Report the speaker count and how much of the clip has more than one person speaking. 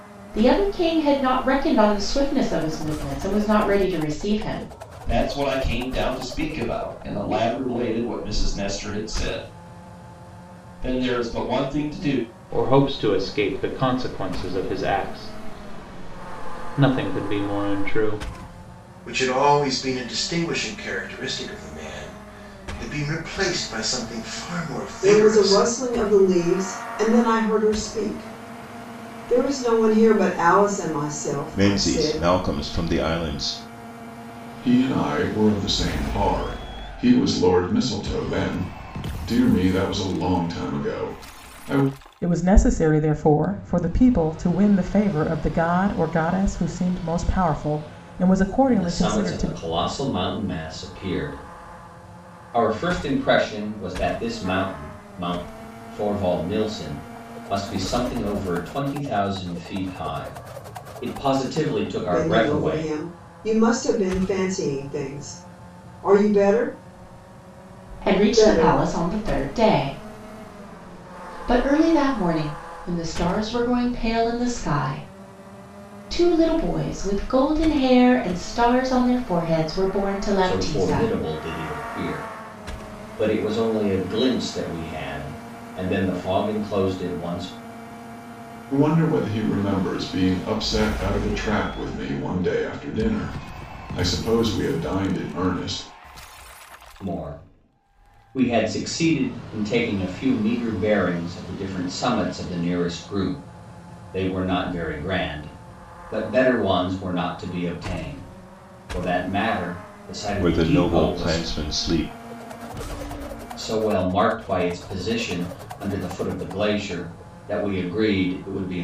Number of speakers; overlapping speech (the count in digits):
9, about 5%